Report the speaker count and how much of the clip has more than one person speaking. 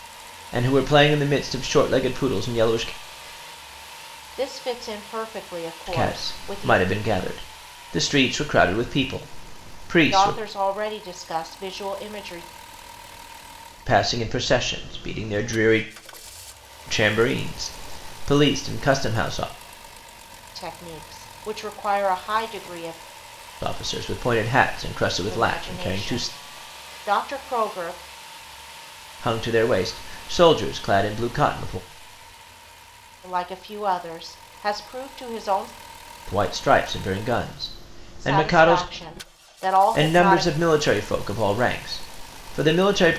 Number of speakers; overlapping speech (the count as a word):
two, about 8%